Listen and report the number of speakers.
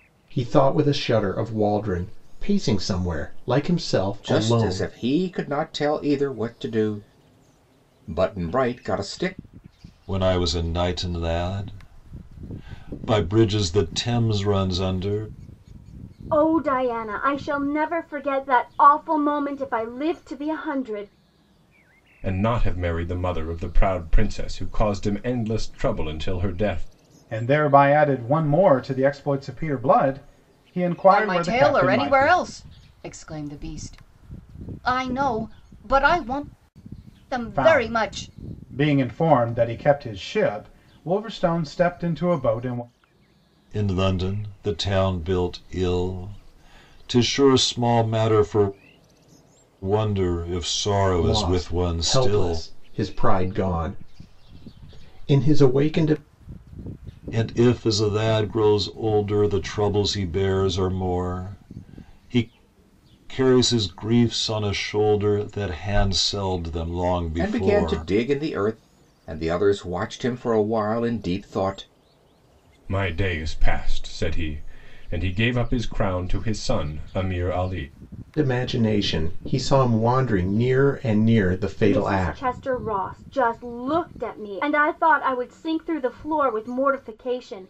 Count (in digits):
7